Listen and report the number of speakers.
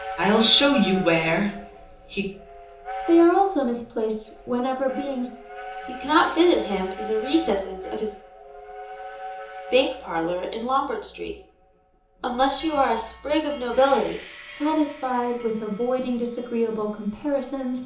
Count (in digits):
3